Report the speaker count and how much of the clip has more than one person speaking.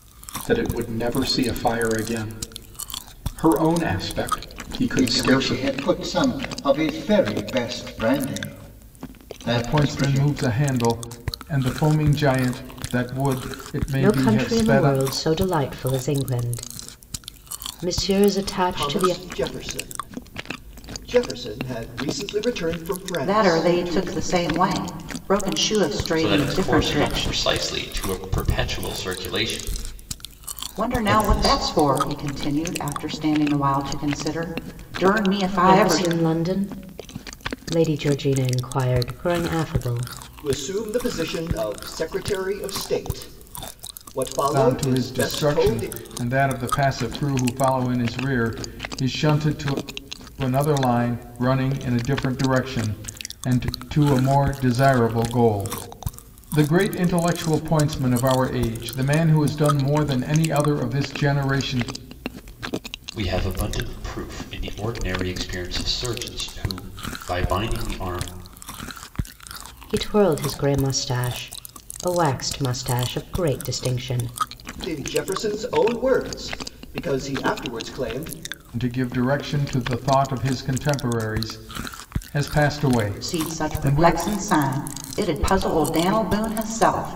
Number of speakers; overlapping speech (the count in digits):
7, about 10%